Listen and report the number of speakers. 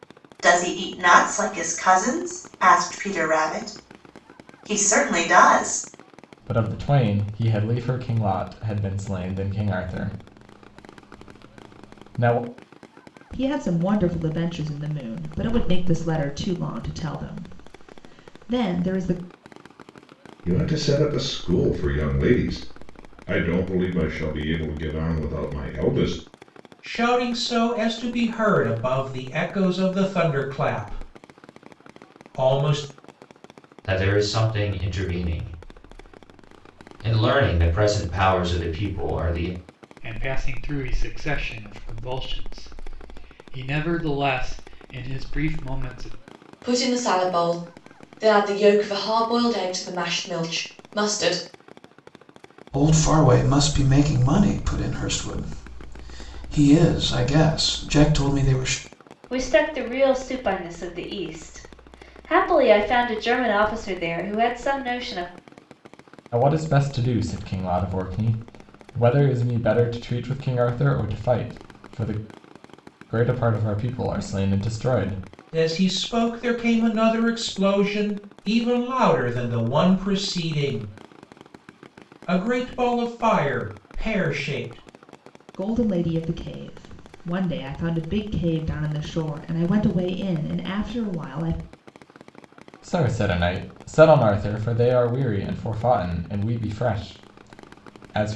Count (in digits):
10